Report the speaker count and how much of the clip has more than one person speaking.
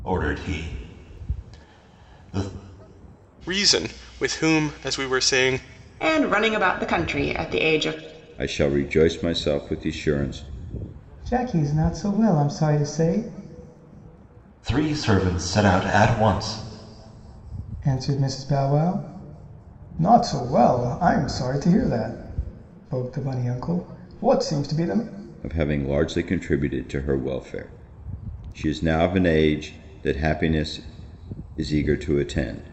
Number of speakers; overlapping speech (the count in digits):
5, no overlap